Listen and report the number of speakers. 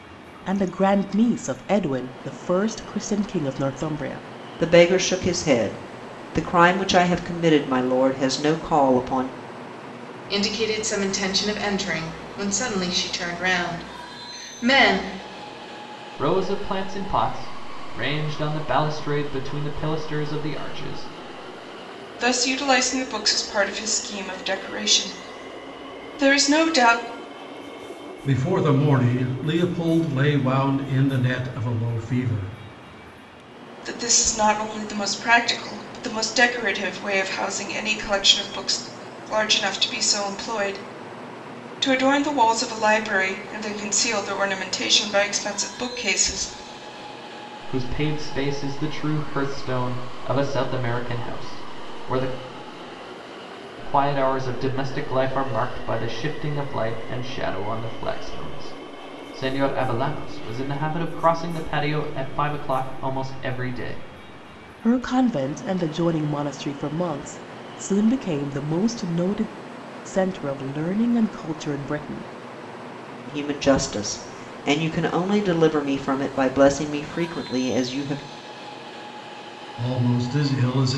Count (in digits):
6